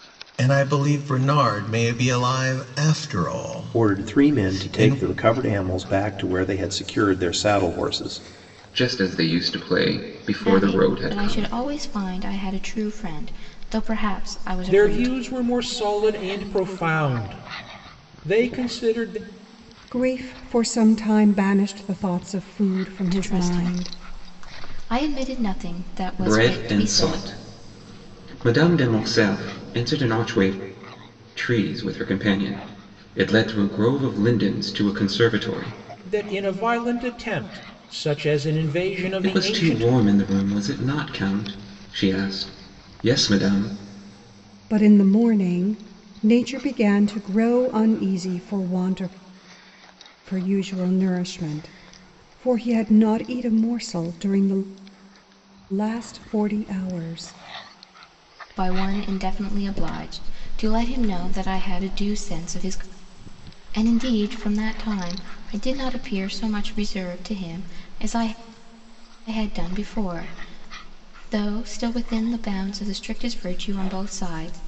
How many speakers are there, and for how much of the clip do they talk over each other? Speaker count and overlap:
6, about 8%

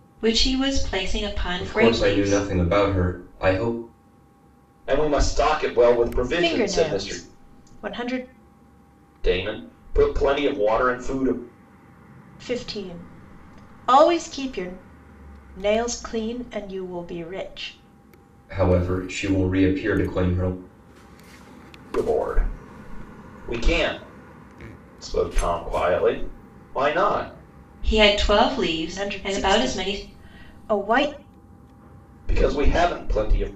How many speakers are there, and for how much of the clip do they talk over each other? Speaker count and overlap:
4, about 9%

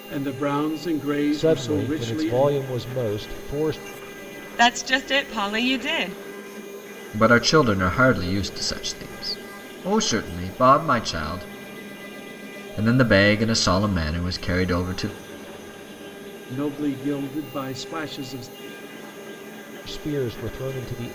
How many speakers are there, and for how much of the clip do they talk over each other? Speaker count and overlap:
4, about 6%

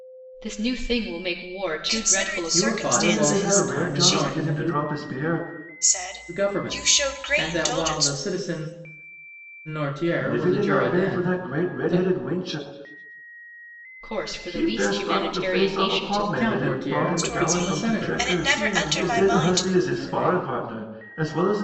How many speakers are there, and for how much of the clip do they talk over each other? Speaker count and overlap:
4, about 59%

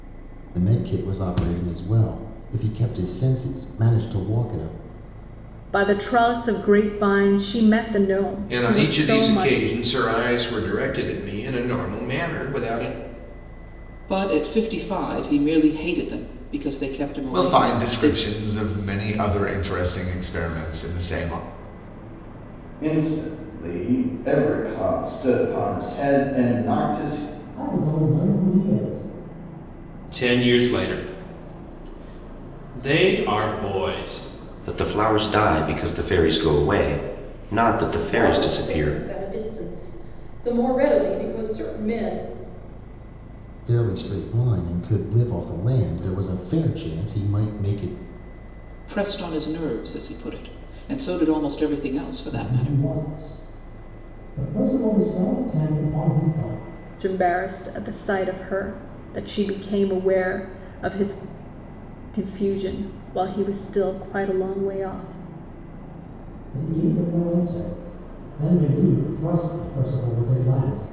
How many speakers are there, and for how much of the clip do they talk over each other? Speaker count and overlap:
10, about 5%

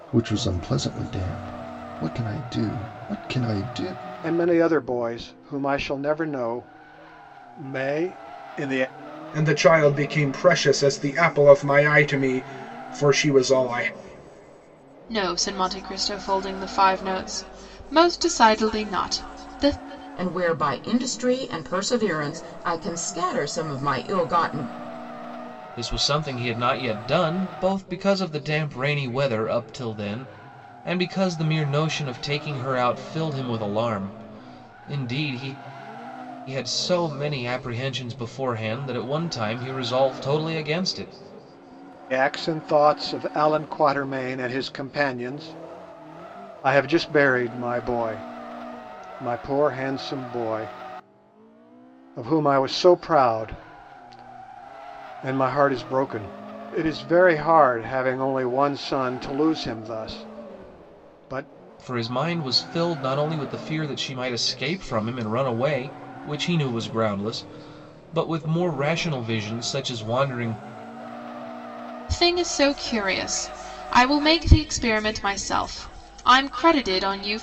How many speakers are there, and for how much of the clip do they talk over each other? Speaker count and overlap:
6, no overlap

